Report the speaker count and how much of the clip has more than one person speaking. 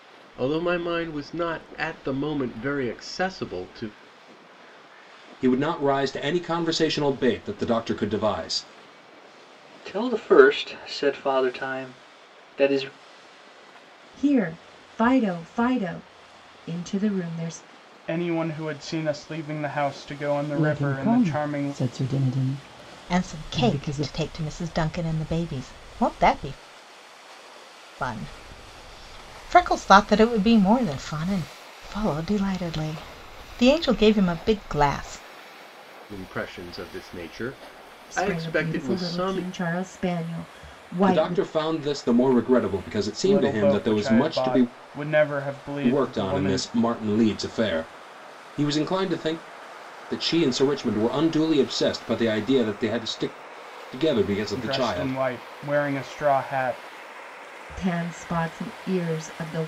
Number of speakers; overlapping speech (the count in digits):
7, about 12%